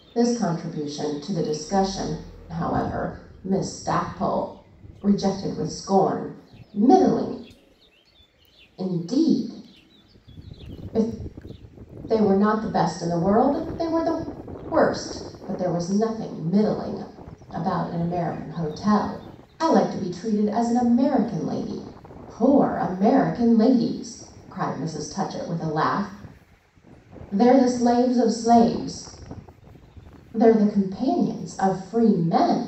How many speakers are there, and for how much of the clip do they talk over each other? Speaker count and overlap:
one, no overlap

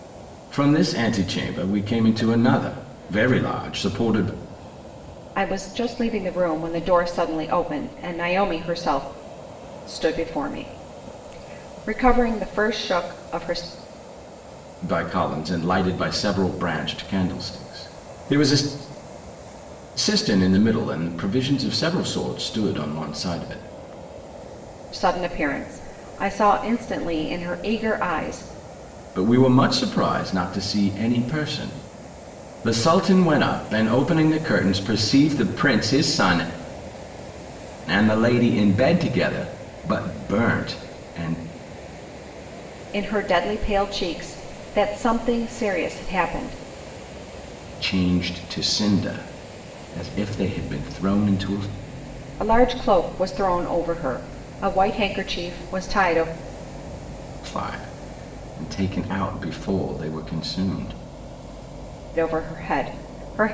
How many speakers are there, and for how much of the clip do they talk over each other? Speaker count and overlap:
two, no overlap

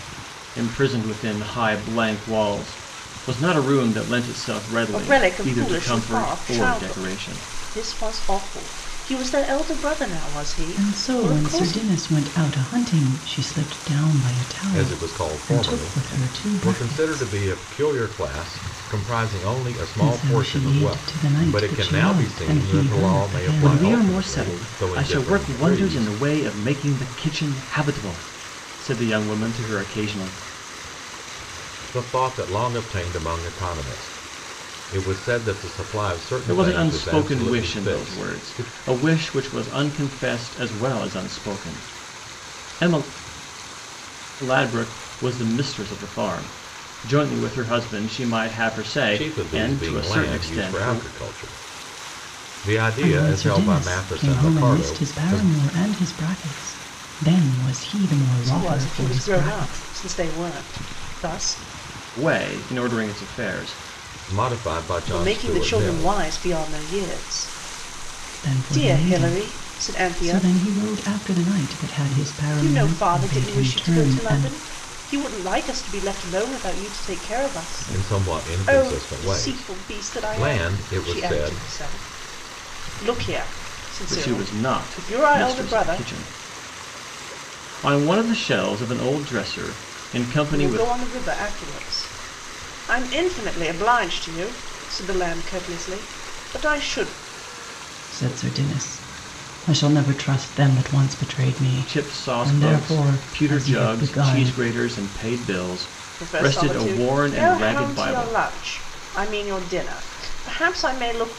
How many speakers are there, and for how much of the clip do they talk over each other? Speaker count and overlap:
four, about 33%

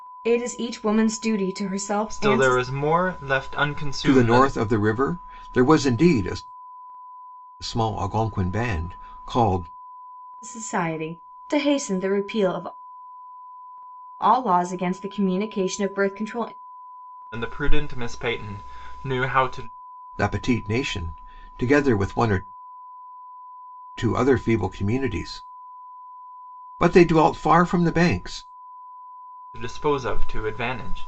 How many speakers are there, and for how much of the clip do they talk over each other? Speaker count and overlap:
three, about 3%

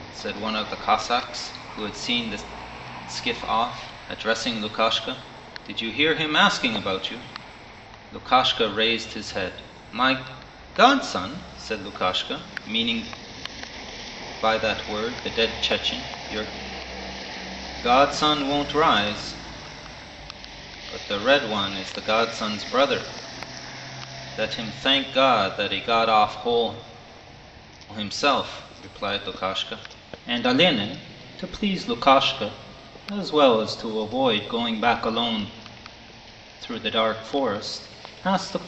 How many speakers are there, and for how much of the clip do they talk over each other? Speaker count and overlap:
one, no overlap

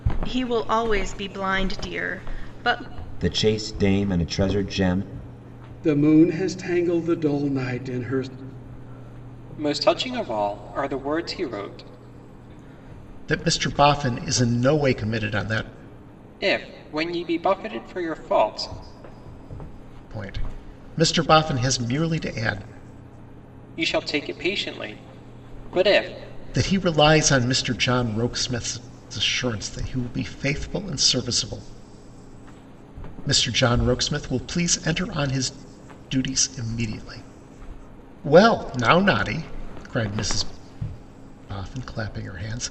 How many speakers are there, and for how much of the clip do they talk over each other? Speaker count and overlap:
five, no overlap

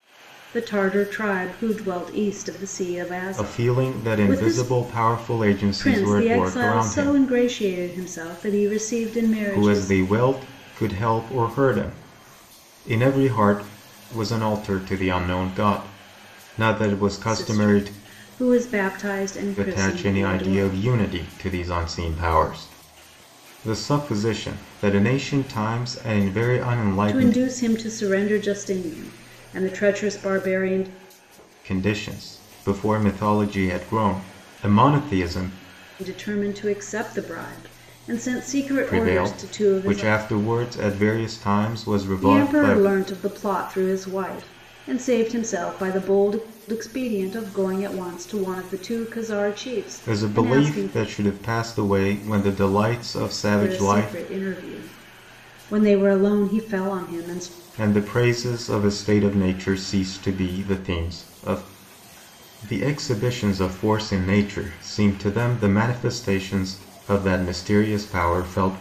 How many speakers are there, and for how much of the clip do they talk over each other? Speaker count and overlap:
two, about 14%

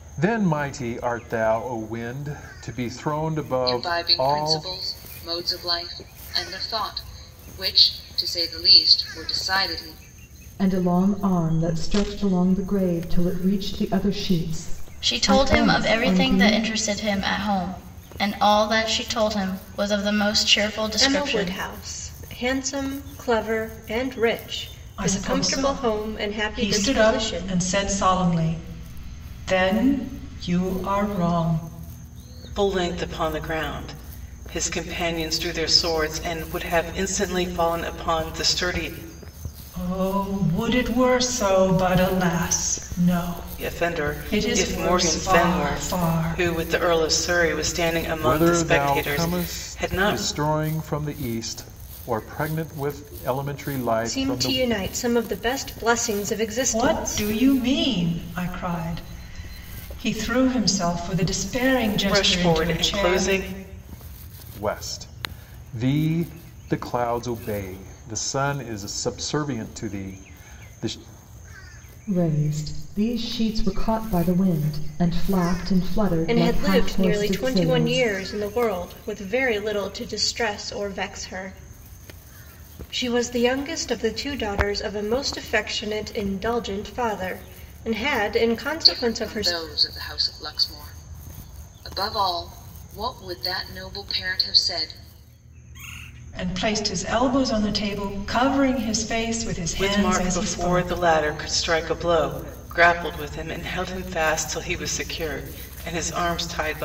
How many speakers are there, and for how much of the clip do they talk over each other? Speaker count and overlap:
seven, about 16%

